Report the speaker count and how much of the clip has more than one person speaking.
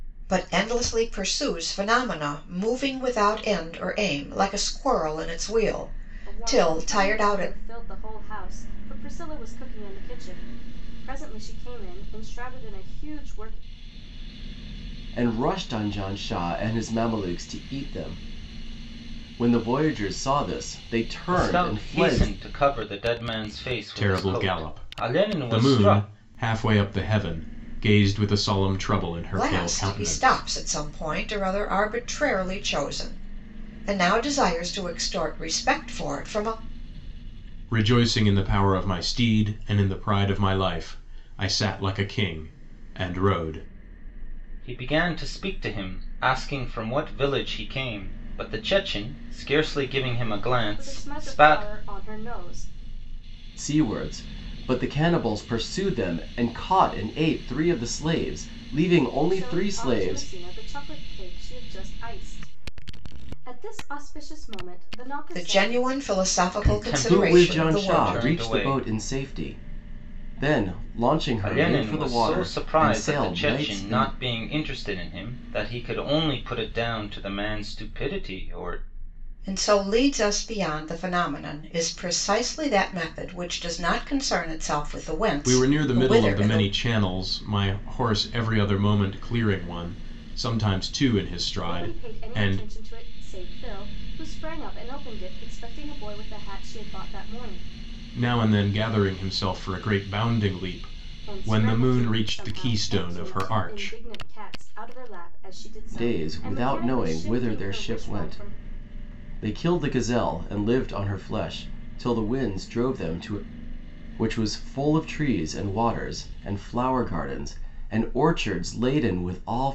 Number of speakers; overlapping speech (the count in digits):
5, about 18%